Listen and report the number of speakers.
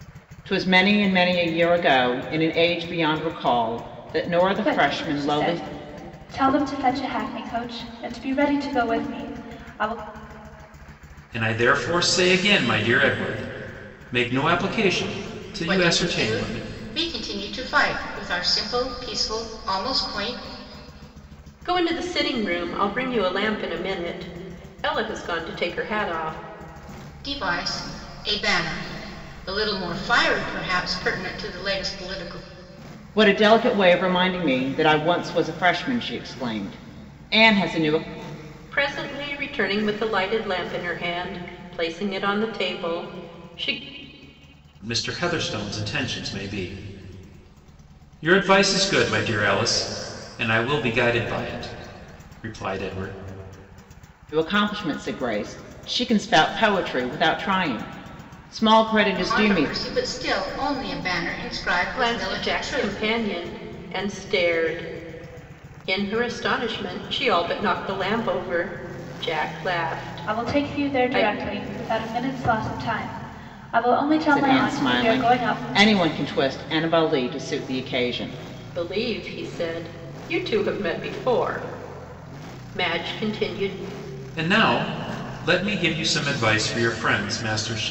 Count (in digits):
5